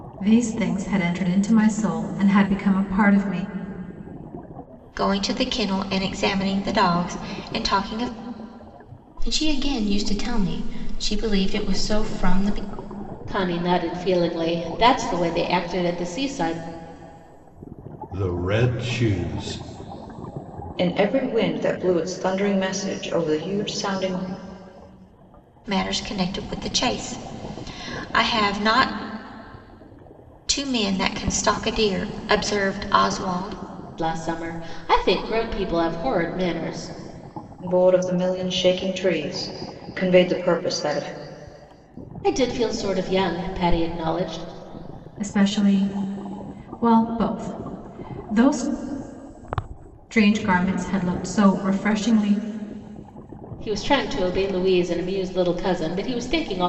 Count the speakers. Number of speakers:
6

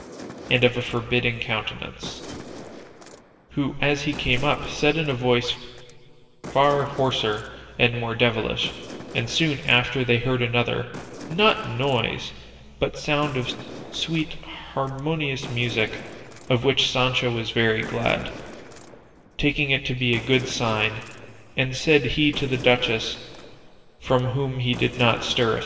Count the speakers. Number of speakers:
1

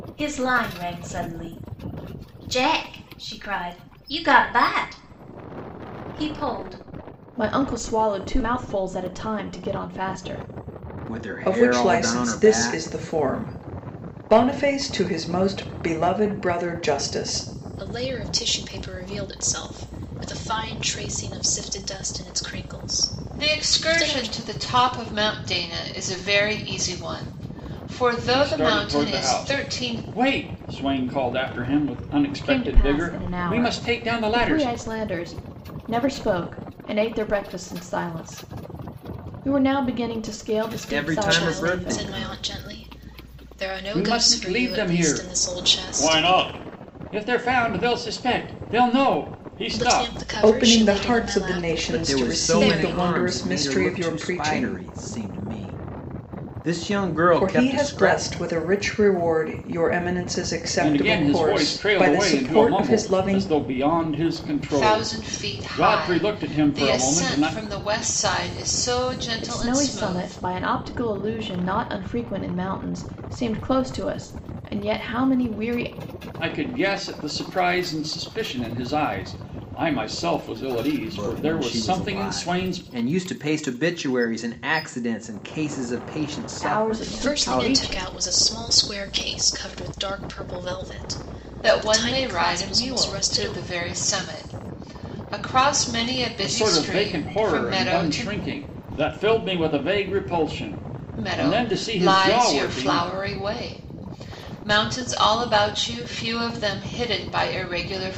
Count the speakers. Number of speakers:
7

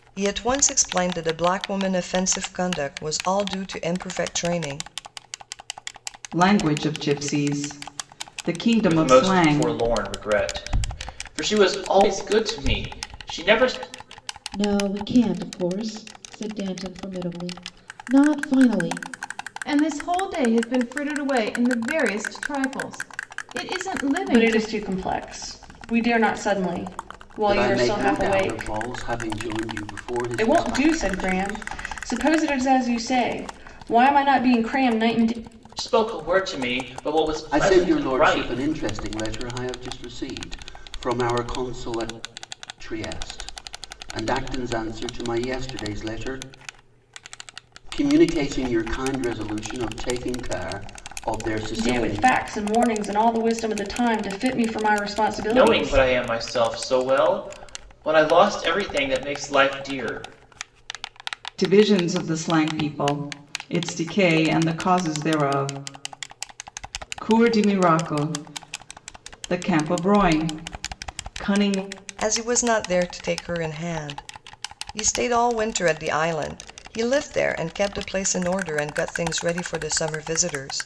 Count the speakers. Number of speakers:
7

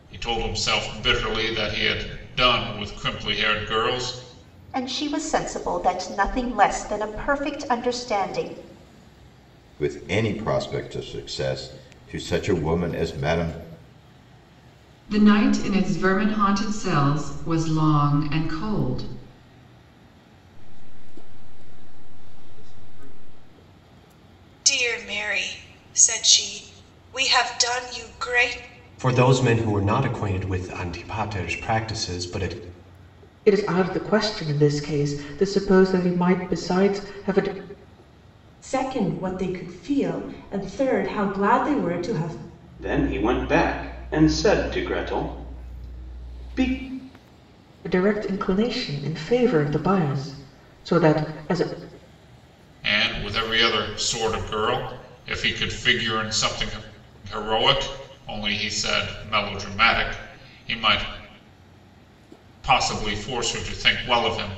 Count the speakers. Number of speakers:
10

